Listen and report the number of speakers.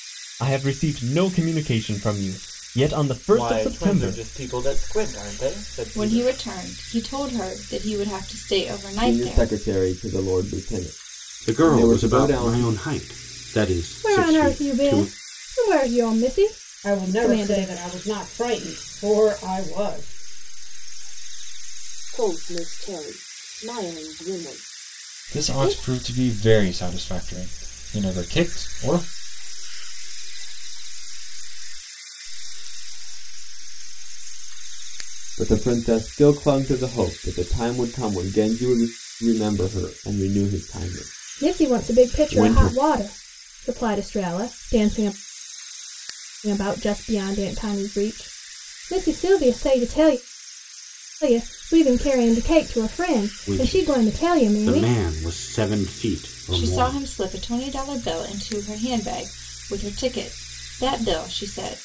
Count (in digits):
10